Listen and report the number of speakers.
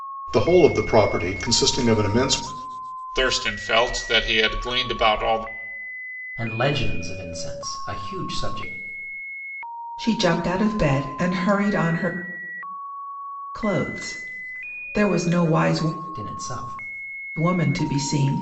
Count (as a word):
four